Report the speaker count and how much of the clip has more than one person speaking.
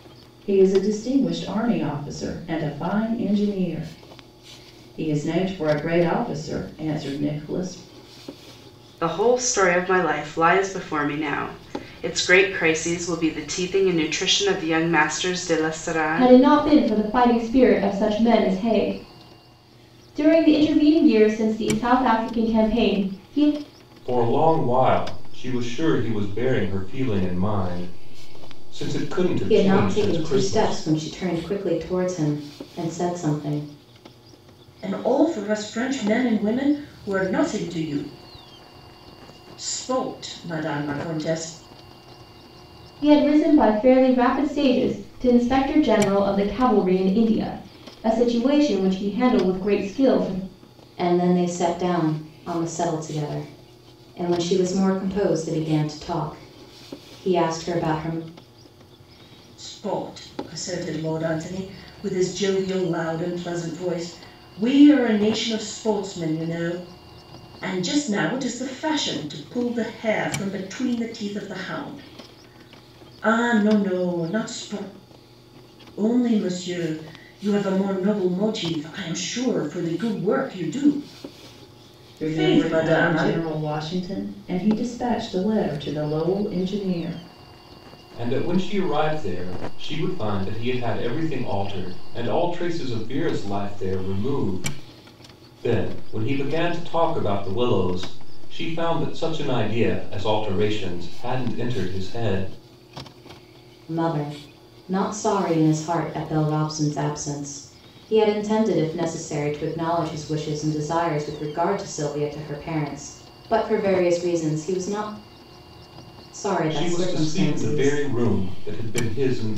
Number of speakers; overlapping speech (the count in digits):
6, about 4%